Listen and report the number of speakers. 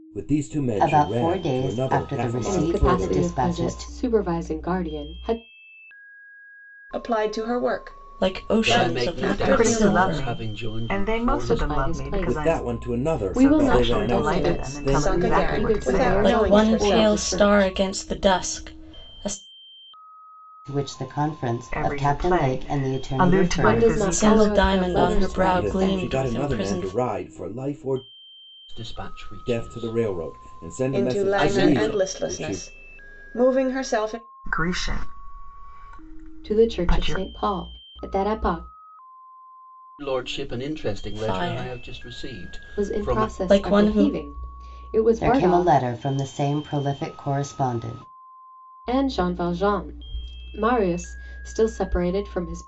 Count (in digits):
7